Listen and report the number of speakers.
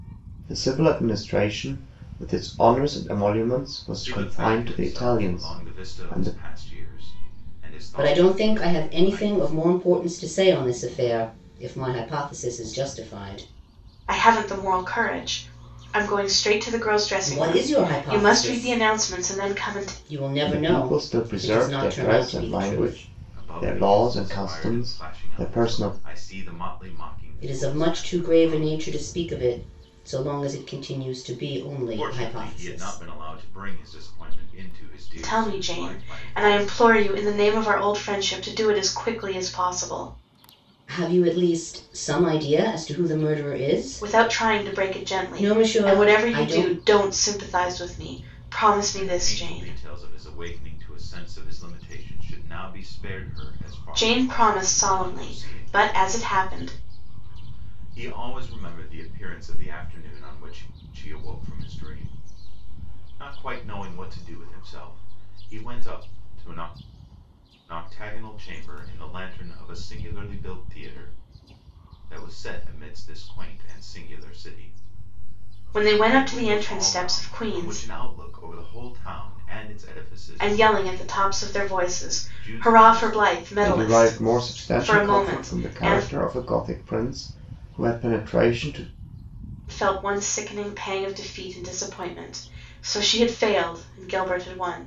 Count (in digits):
4